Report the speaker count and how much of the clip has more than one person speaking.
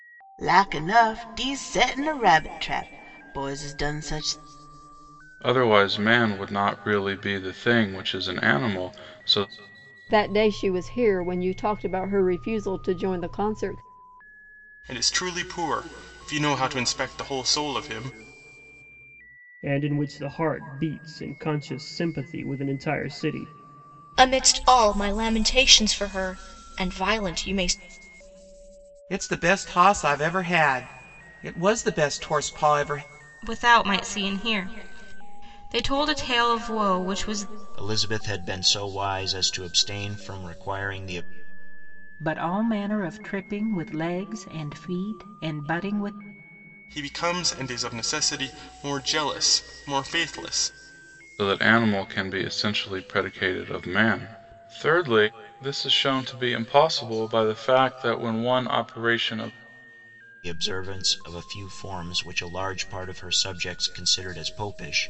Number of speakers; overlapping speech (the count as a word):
ten, no overlap